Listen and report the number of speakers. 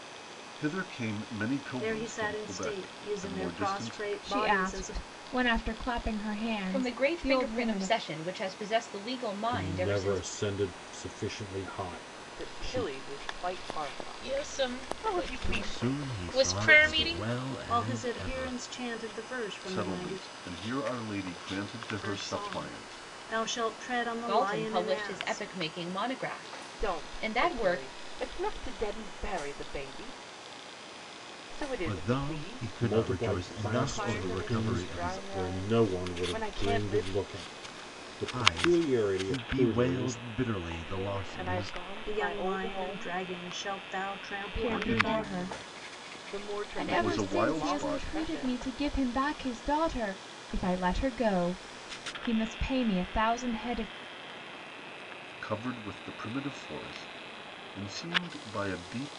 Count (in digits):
8